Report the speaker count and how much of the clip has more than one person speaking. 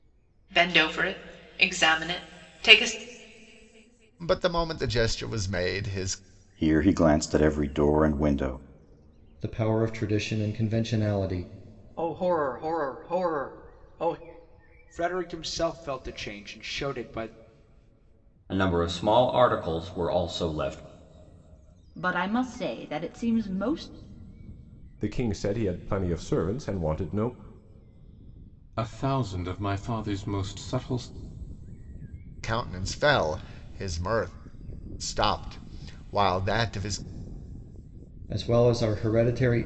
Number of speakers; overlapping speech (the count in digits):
10, no overlap